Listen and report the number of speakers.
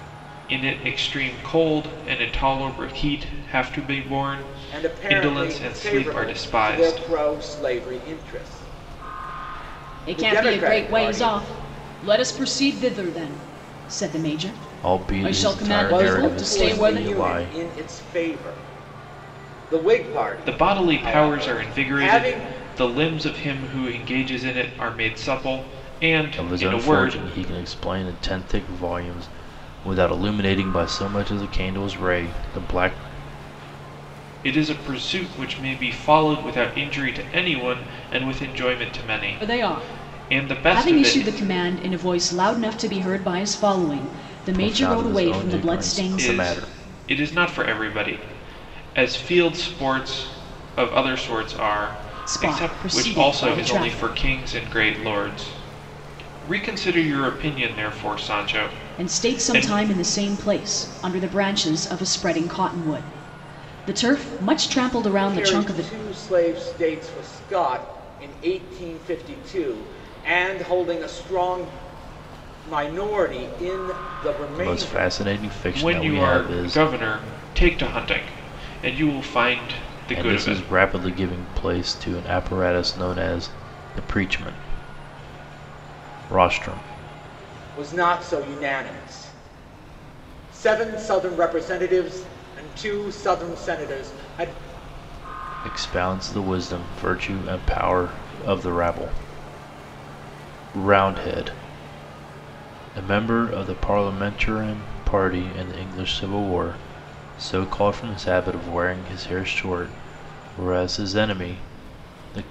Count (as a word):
four